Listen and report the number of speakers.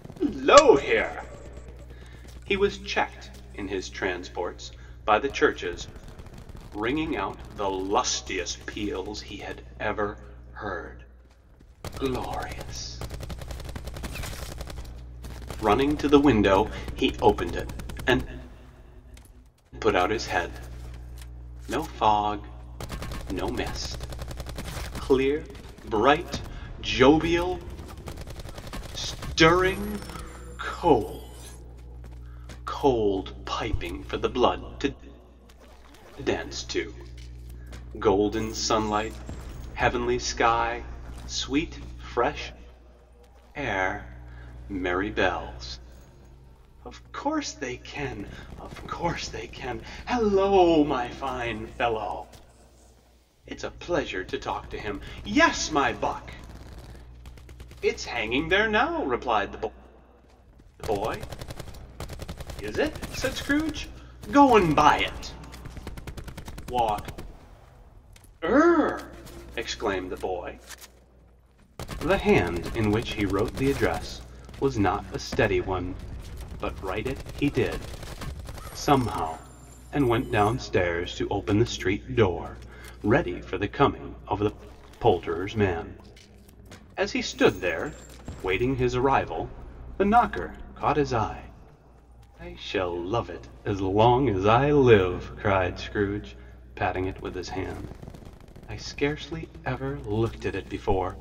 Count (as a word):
one